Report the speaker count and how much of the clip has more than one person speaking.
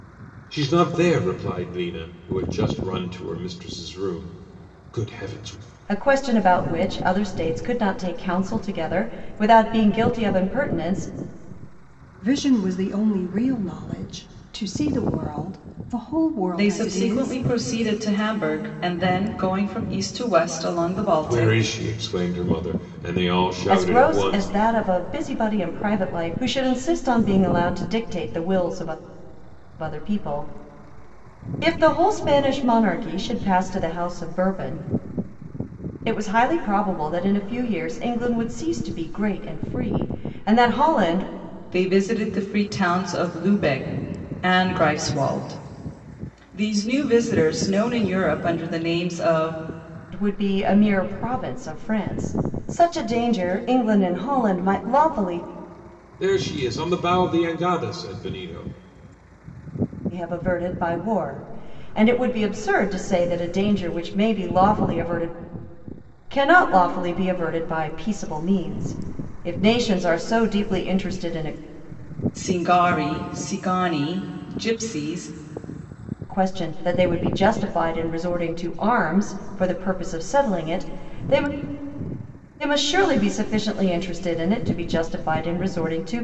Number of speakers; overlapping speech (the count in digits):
4, about 3%